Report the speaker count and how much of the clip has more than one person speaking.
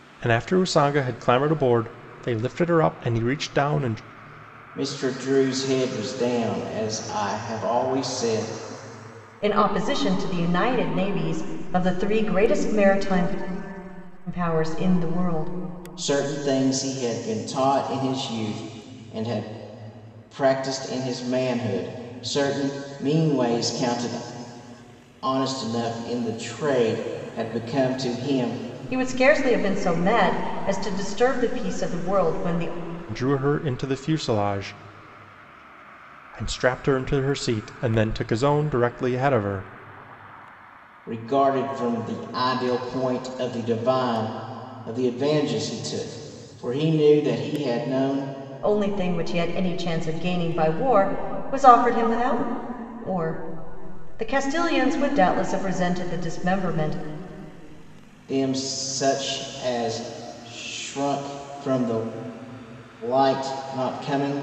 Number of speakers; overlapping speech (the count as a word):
three, no overlap